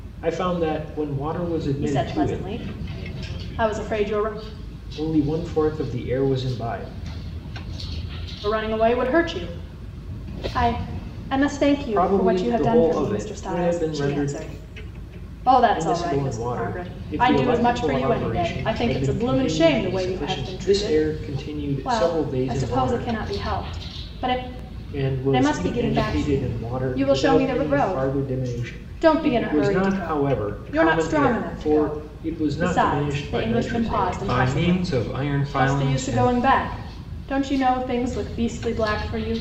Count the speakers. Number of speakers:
two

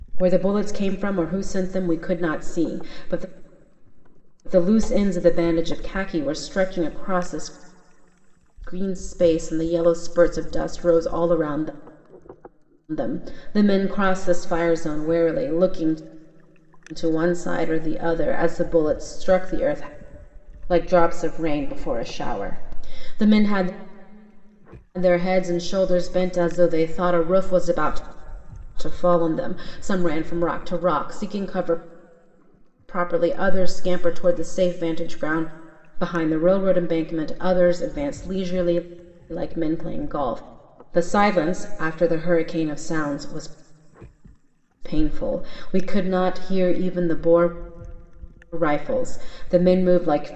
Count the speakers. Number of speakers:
one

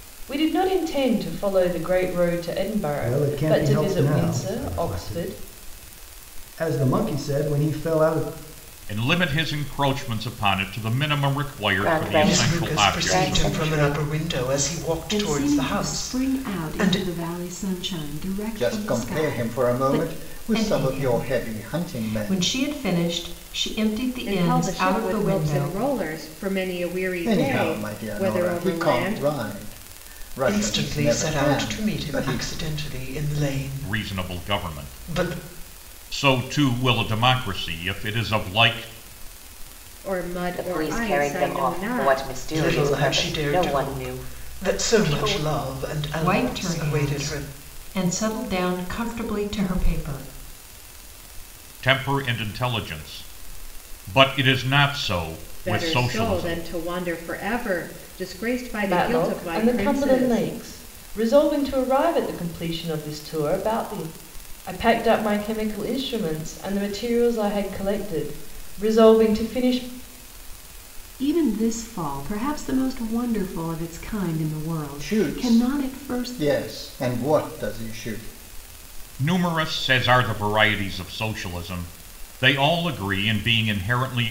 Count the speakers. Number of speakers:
nine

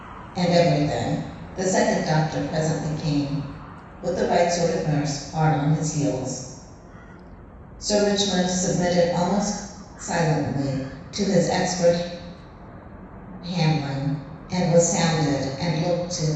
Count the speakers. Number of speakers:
one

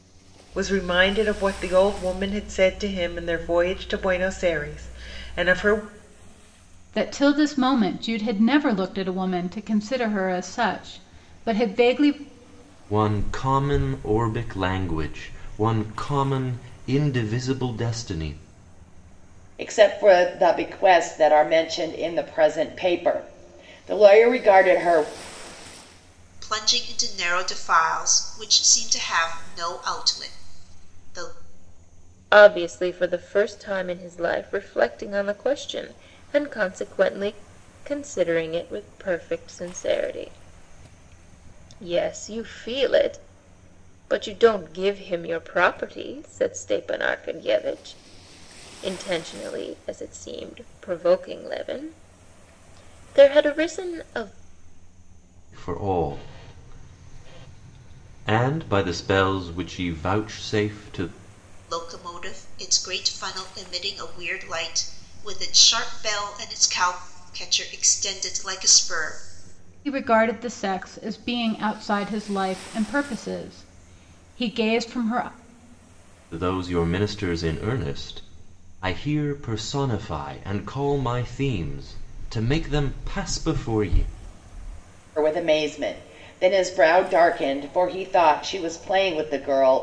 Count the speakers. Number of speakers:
six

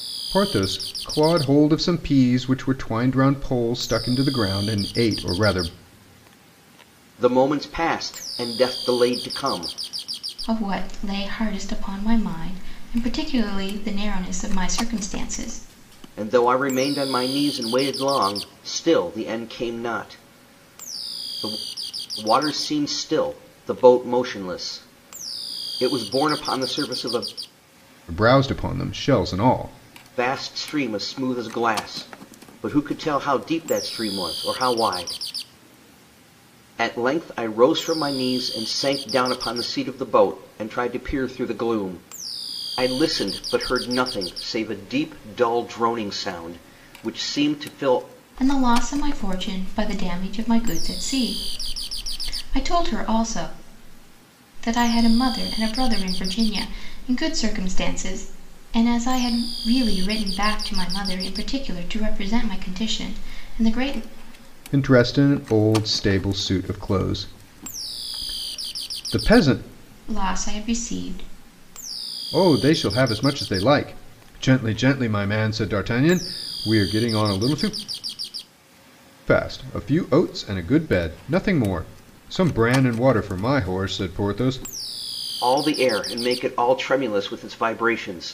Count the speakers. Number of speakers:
three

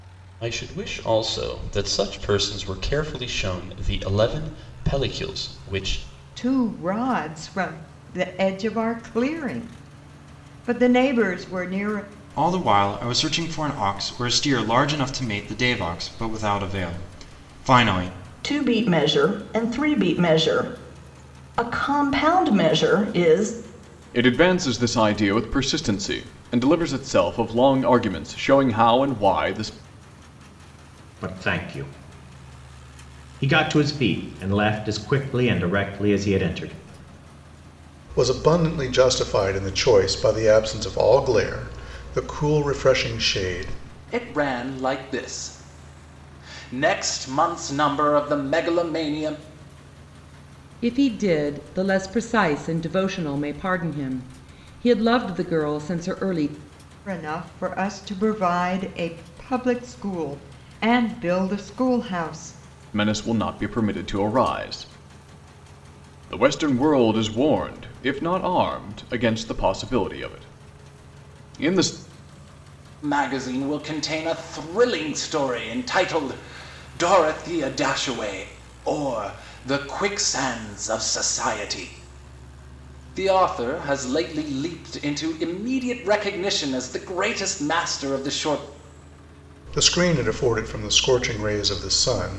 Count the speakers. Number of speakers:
nine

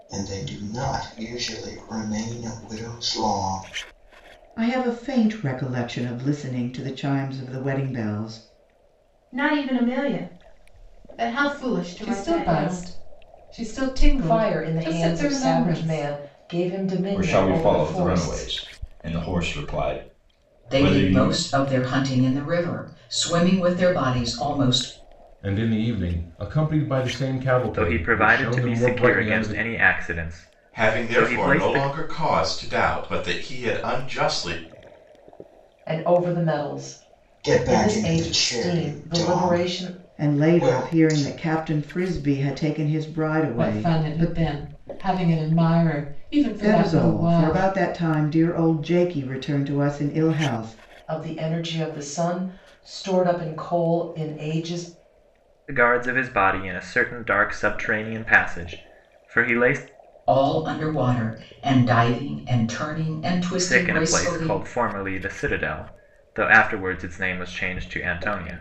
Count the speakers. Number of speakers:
ten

